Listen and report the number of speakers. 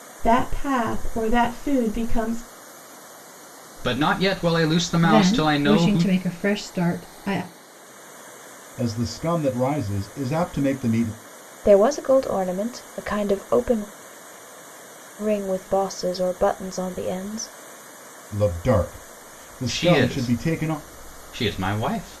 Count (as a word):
five